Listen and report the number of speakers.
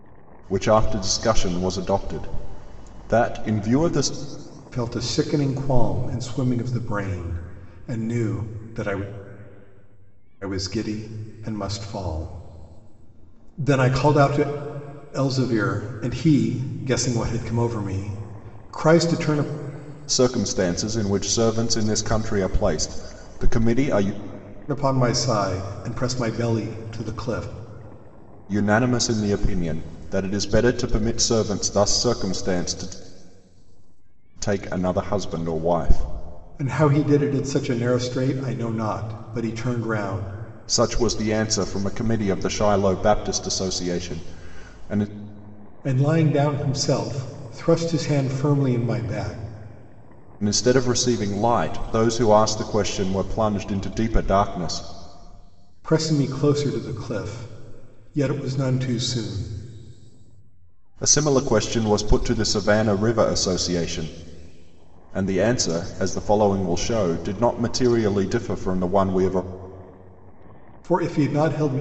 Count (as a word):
two